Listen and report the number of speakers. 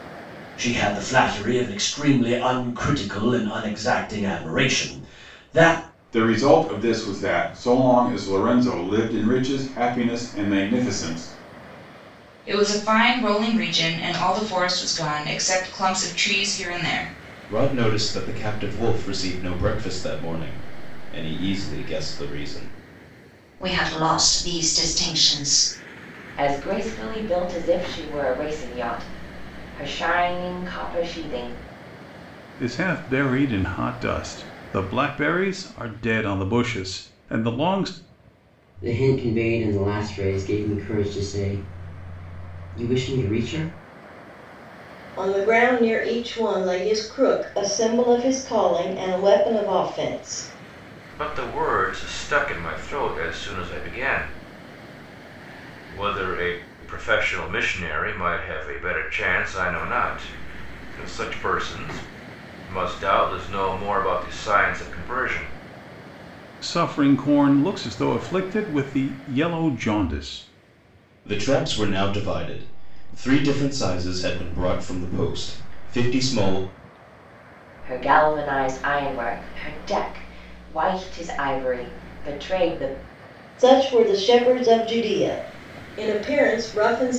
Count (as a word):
ten